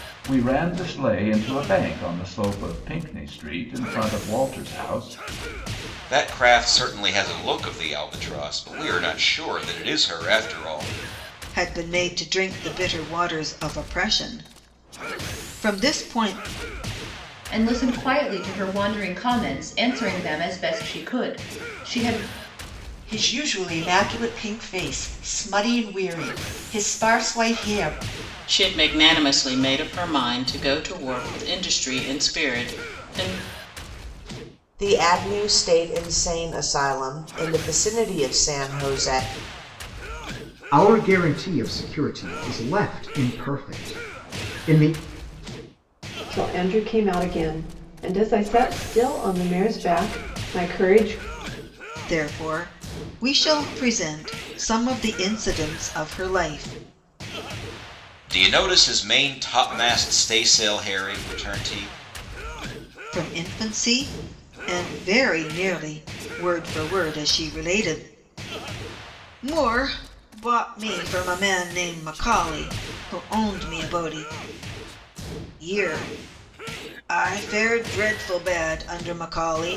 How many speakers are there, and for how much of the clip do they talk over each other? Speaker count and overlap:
nine, no overlap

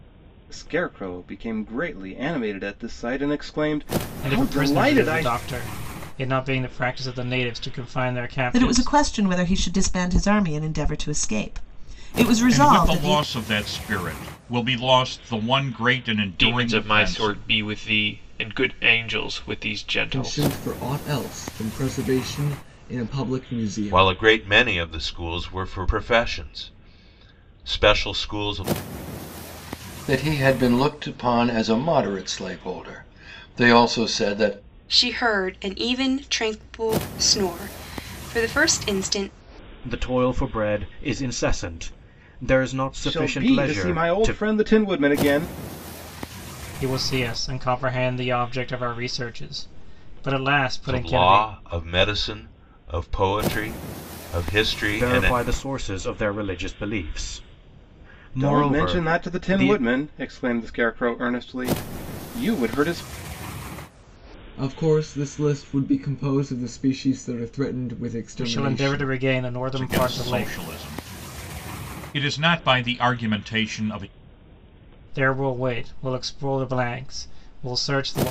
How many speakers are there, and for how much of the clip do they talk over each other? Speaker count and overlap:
ten, about 12%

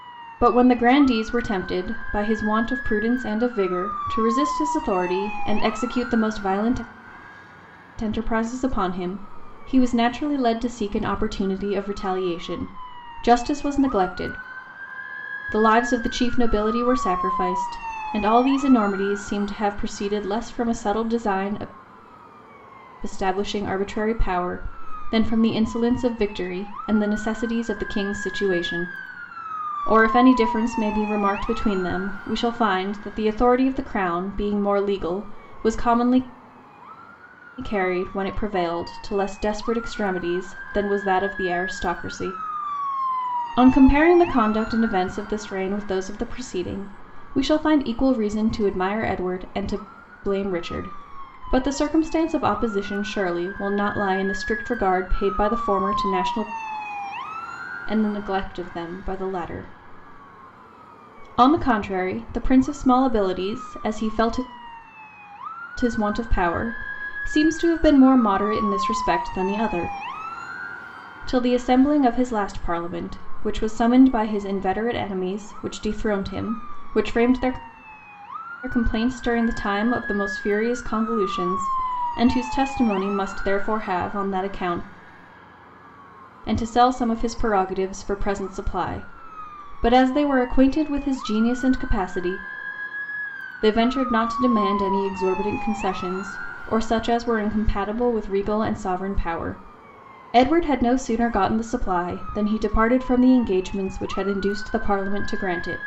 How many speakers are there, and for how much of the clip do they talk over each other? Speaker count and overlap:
one, no overlap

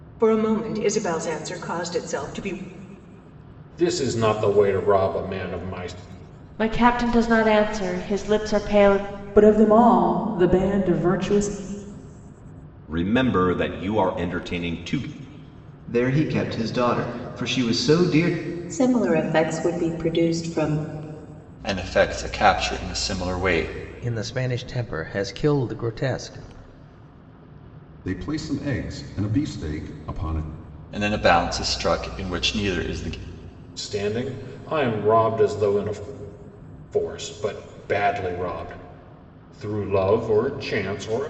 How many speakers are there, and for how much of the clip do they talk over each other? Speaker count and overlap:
ten, no overlap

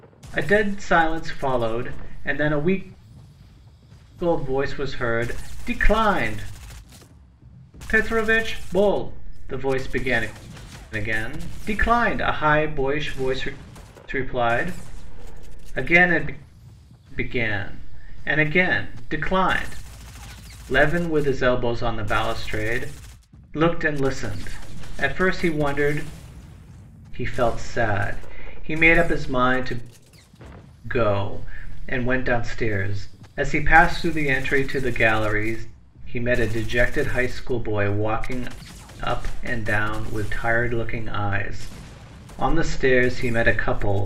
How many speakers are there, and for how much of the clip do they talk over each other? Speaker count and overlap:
one, no overlap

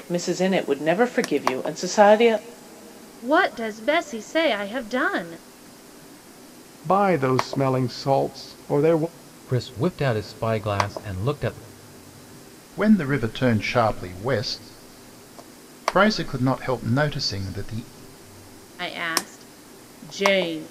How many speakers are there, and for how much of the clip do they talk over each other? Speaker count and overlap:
five, no overlap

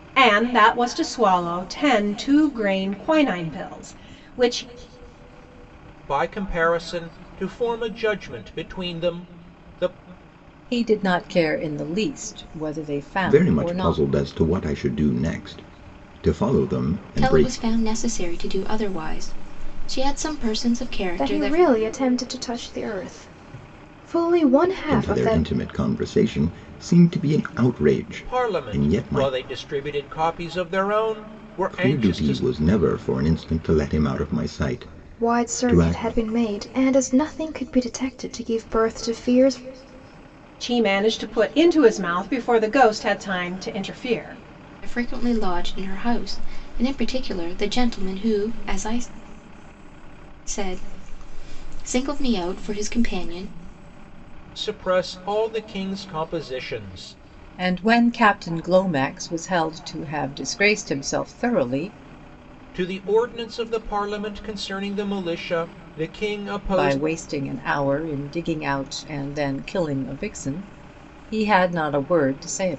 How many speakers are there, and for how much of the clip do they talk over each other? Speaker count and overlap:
six, about 8%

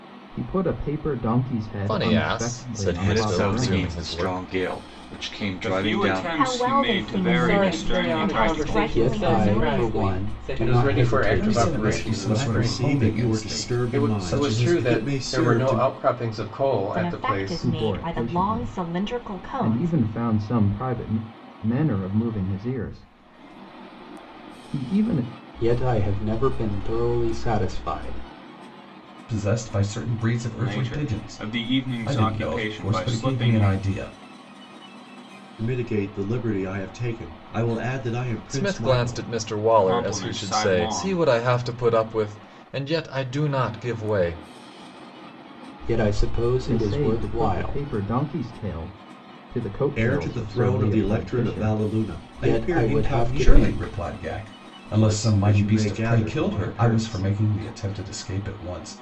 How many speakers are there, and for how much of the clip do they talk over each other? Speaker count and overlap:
ten, about 50%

